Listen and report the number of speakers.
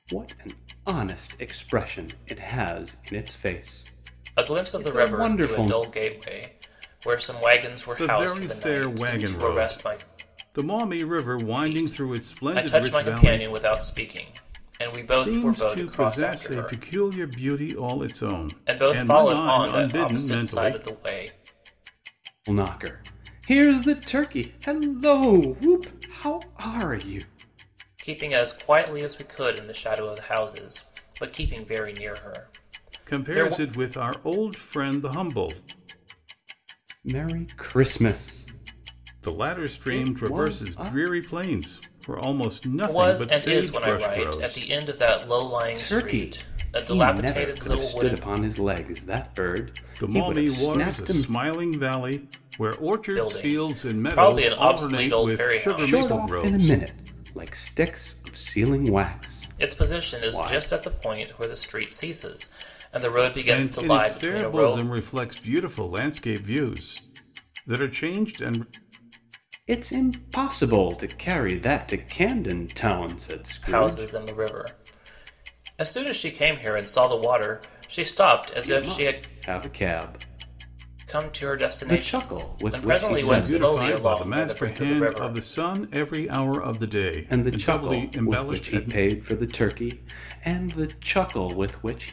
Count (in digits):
3